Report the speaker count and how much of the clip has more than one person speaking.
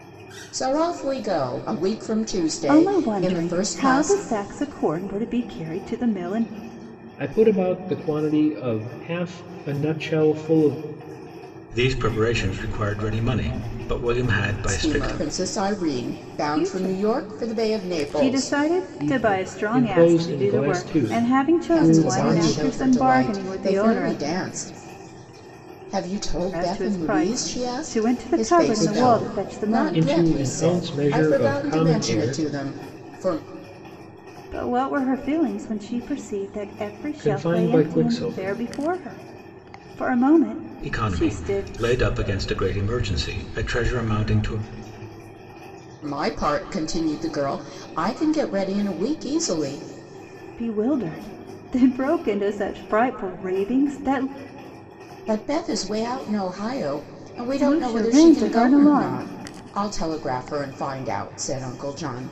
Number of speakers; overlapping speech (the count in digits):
4, about 31%